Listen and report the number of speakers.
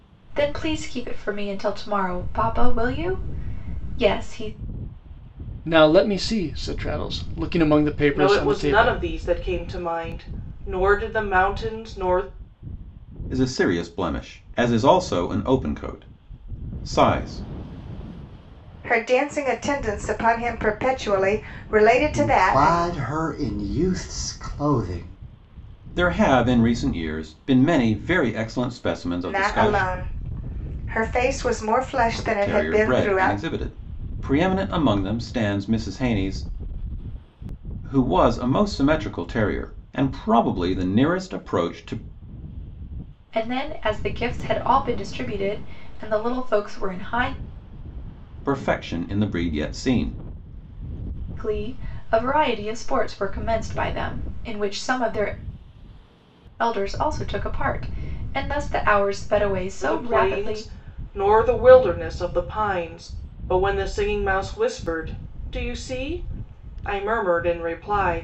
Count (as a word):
six